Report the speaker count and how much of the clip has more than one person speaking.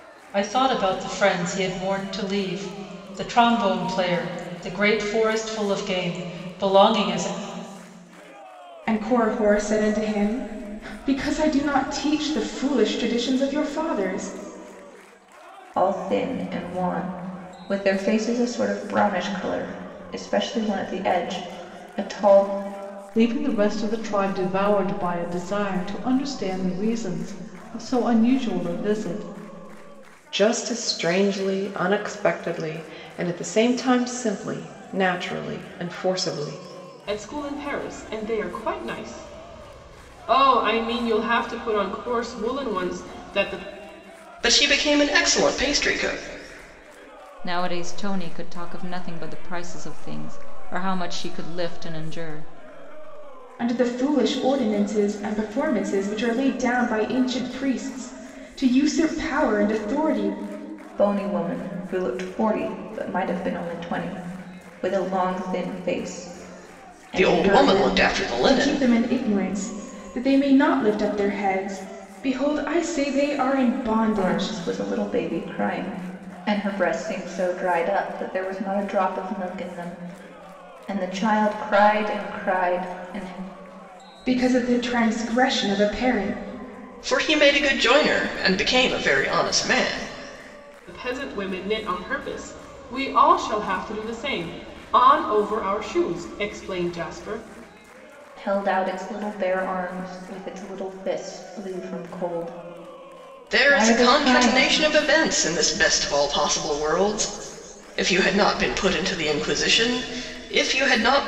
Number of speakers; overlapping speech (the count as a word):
eight, about 3%